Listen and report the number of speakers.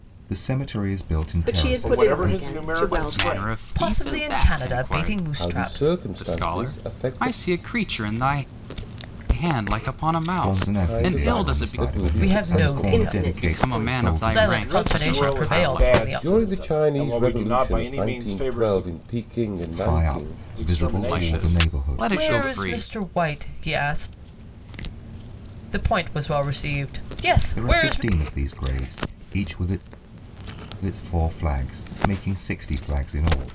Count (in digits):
6